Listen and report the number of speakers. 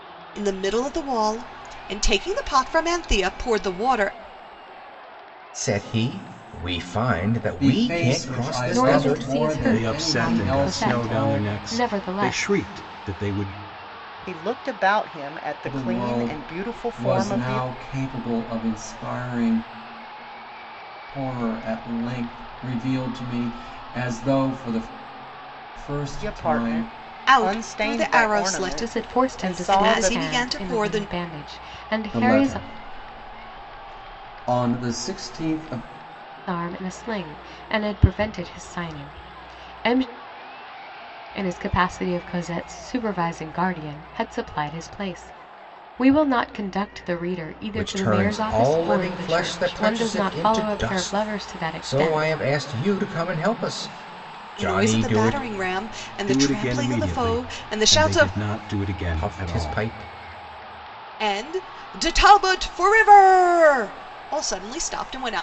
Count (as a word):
six